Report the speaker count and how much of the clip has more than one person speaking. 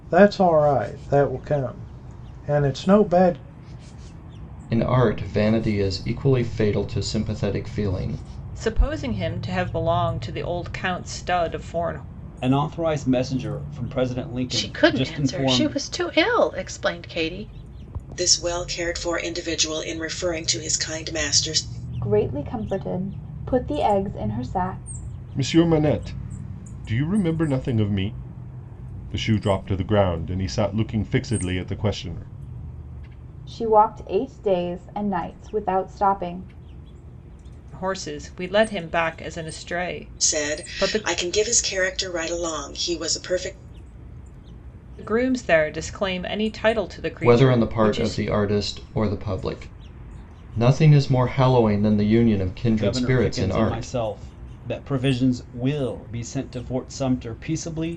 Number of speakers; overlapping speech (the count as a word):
eight, about 8%